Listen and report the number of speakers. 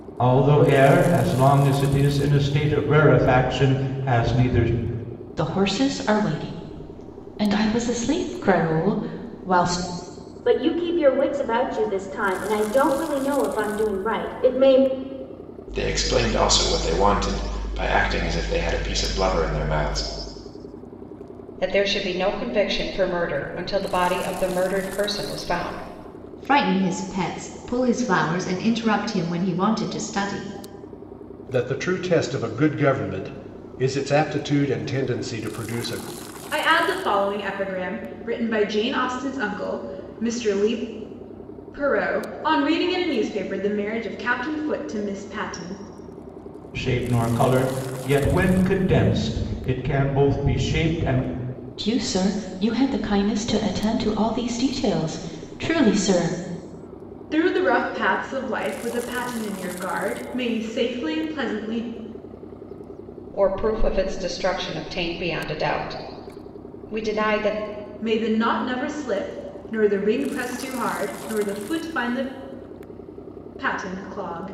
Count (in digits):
8